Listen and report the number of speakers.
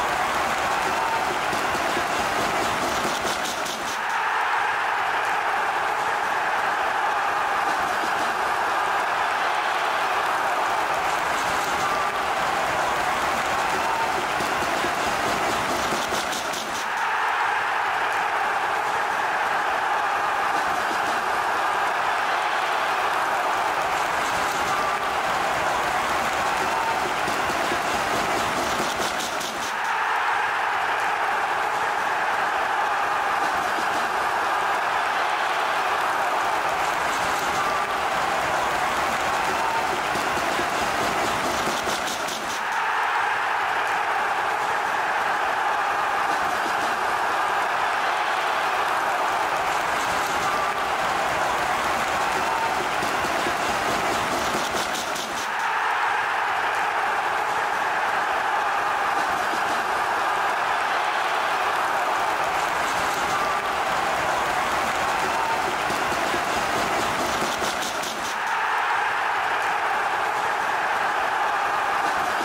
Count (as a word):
zero